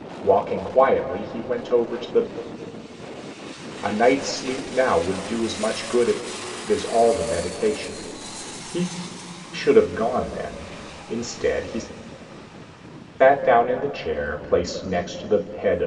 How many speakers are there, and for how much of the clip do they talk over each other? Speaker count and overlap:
one, no overlap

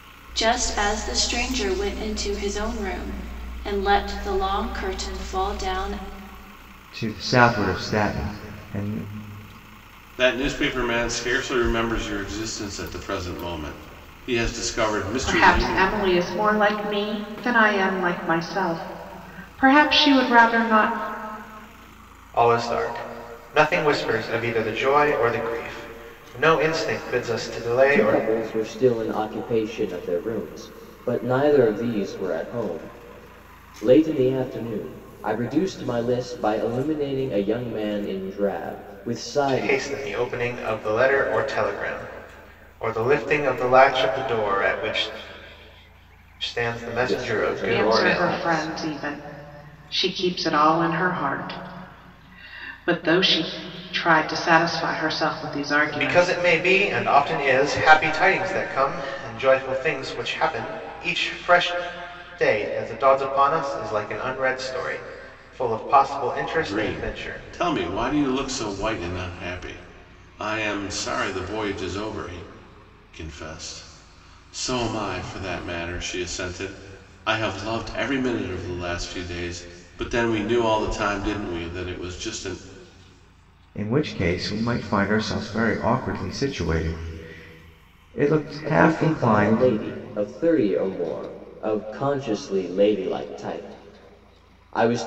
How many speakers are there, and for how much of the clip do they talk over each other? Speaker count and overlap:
six, about 6%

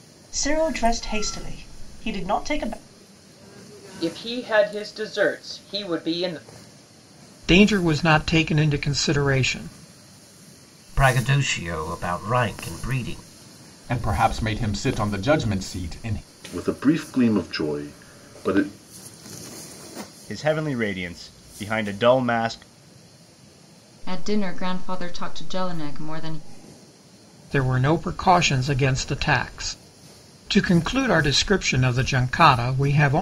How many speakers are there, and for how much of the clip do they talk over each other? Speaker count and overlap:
eight, no overlap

